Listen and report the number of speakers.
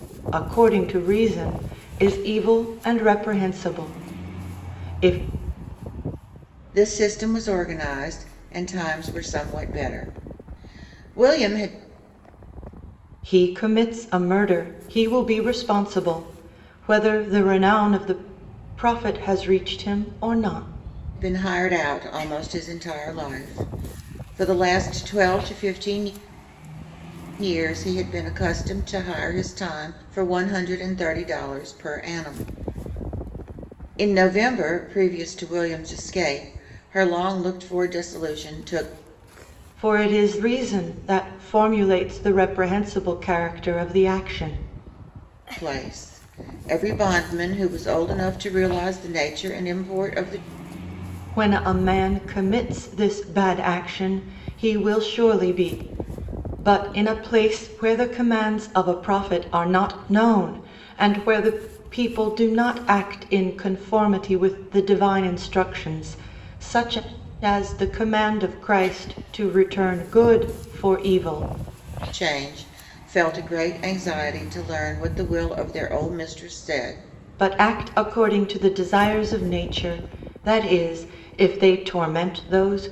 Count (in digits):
2